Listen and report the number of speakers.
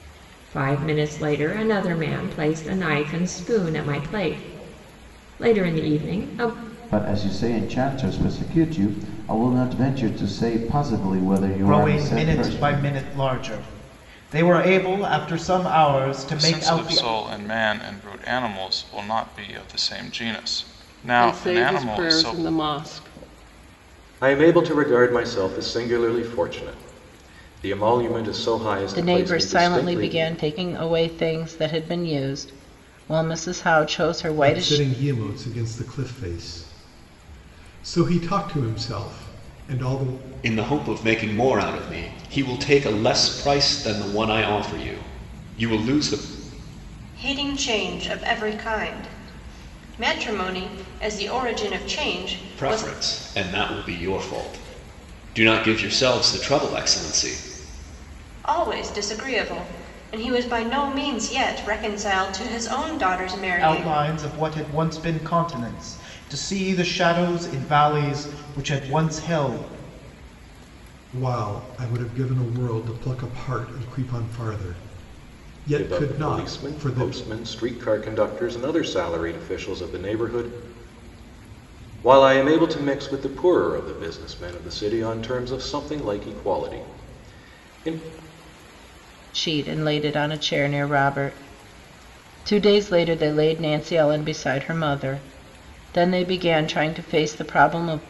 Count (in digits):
10